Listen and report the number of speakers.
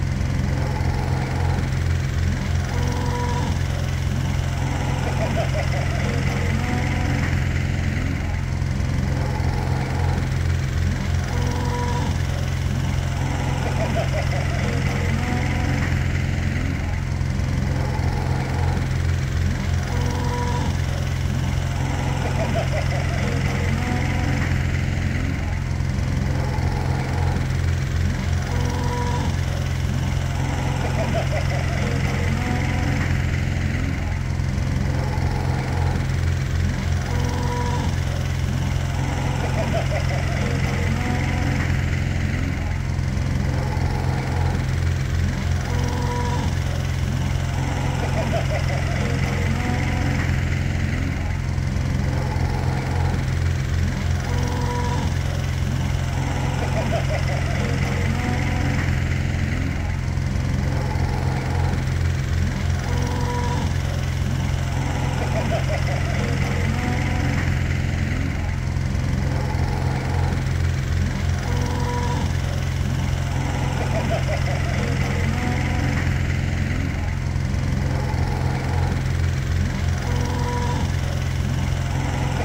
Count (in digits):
0